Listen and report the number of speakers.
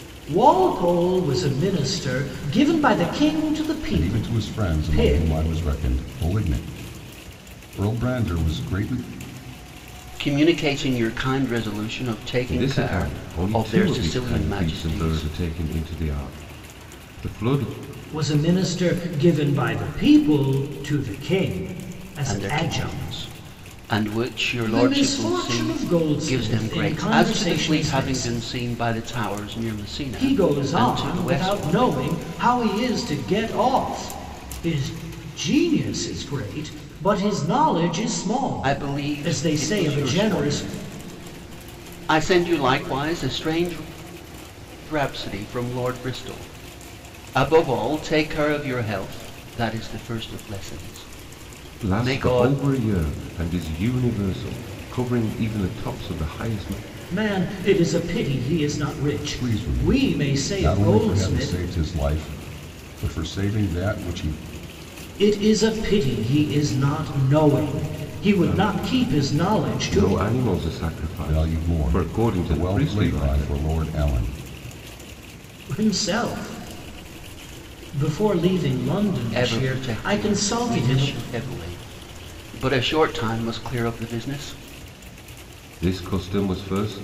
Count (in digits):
4